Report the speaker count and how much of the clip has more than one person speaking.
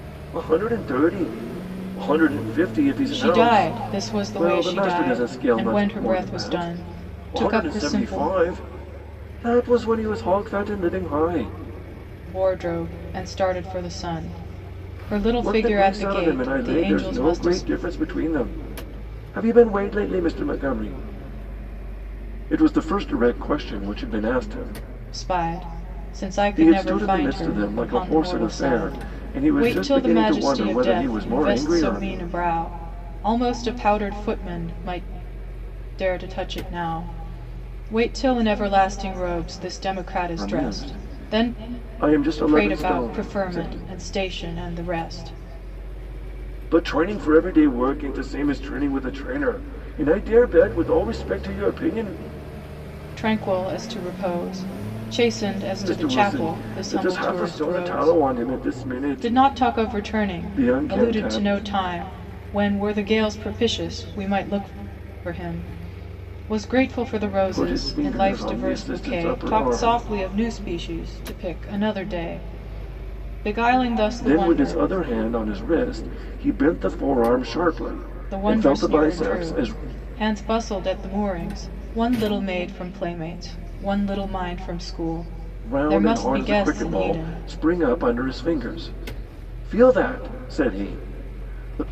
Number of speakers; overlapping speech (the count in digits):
2, about 29%